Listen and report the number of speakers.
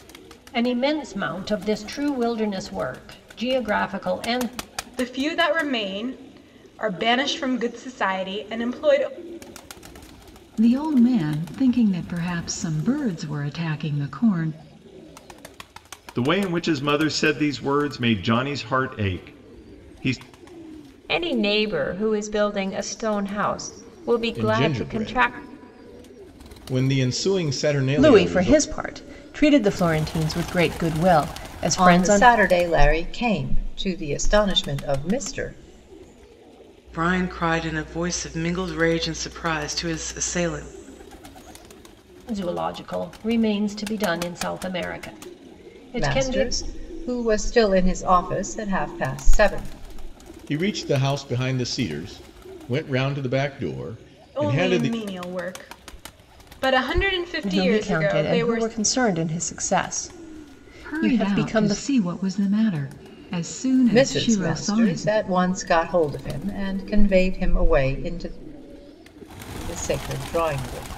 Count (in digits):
9